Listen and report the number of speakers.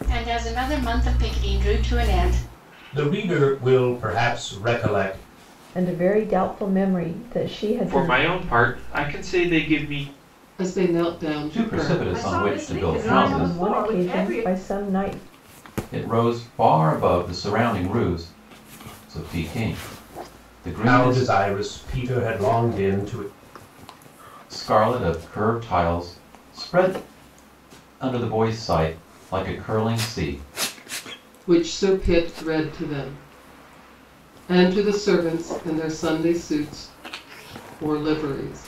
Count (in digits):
7